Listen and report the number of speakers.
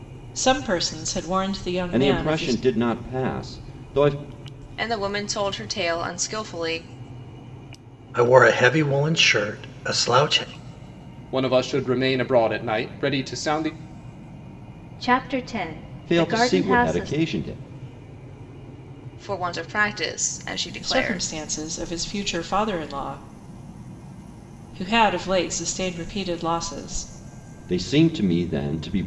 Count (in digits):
6